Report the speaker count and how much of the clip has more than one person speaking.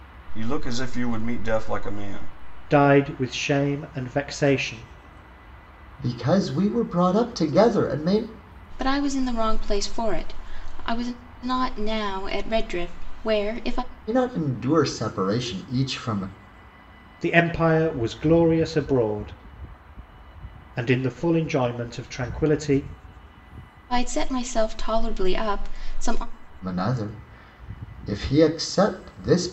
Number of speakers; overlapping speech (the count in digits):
4, no overlap